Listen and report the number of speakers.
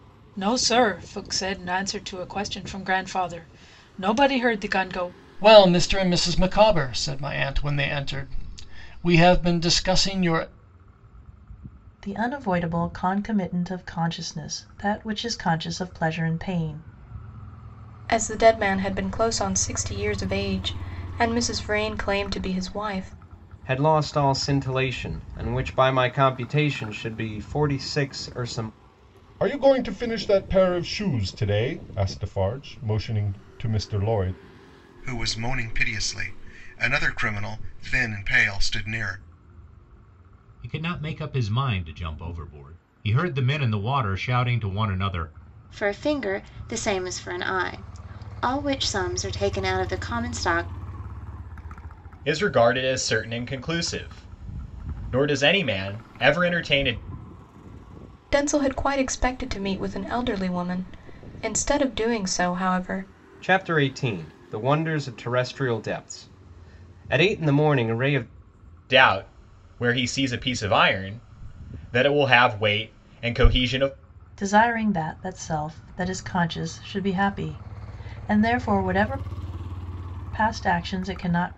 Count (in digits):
10